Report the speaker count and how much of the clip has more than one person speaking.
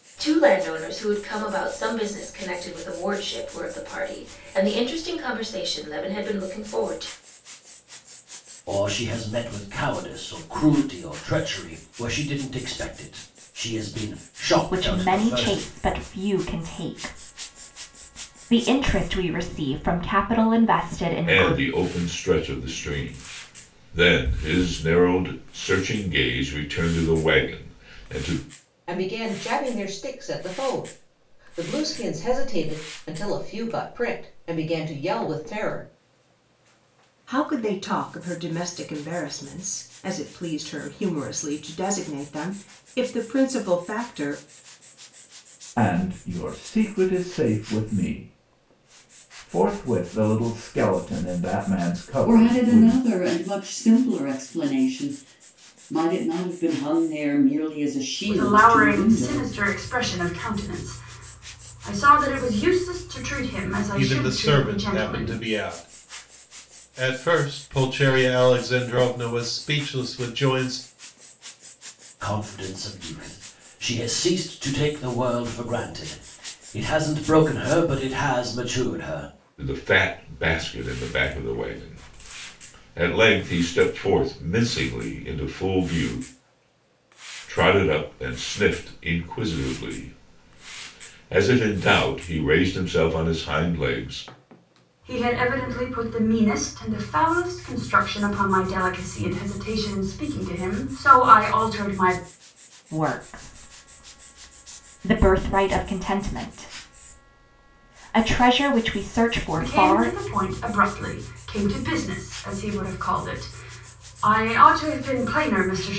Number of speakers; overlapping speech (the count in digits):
10, about 5%